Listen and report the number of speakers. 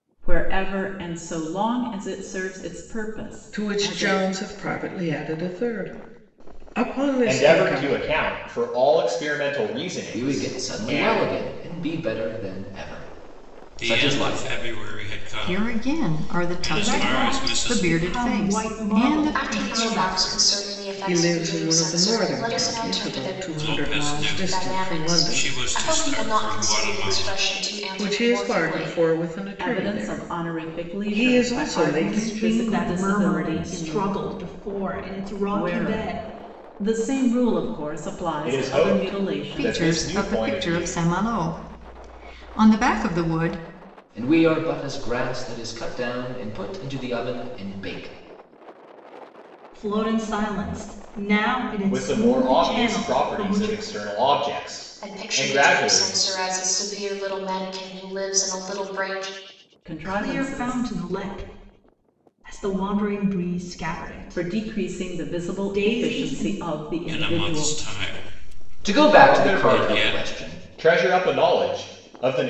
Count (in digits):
8